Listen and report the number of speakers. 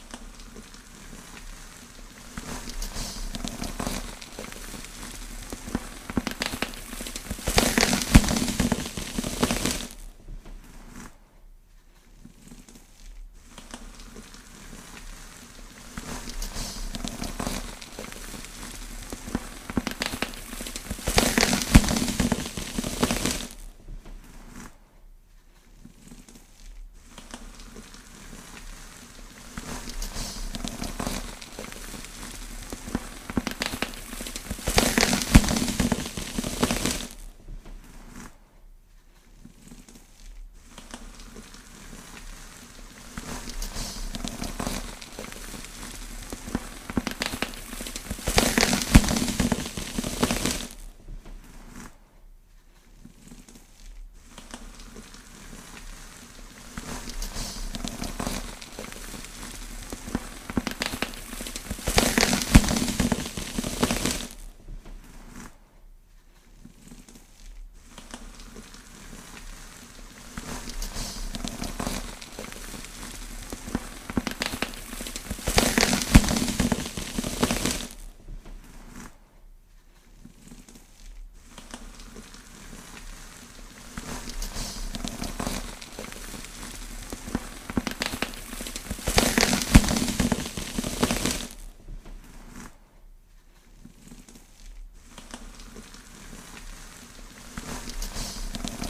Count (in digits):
0